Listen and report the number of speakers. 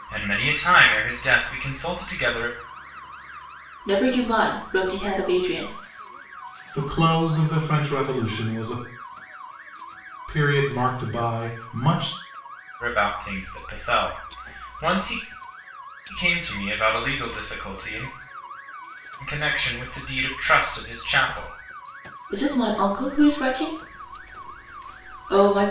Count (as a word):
three